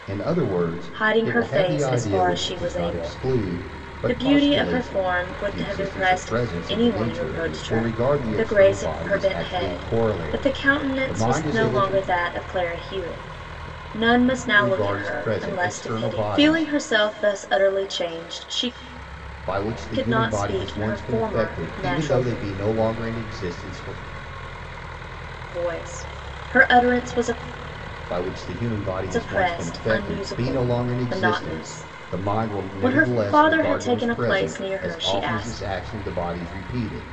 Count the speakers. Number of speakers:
two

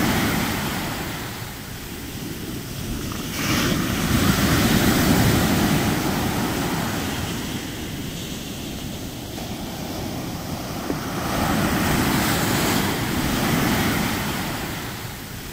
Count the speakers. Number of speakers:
zero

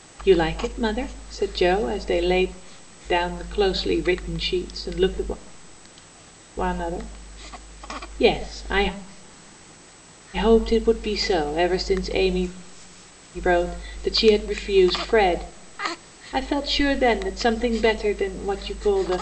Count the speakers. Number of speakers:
one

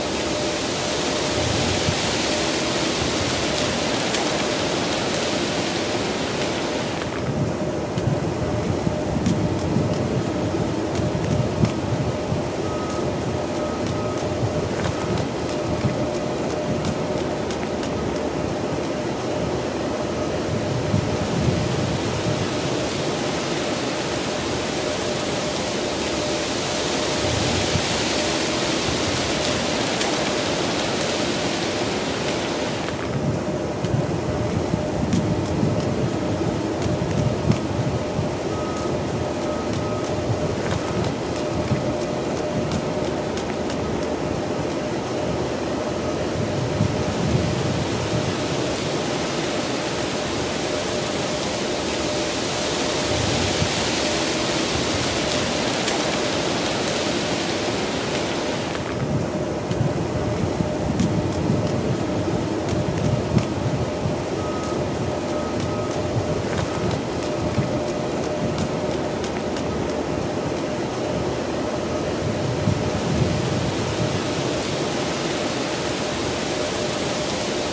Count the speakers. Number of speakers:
zero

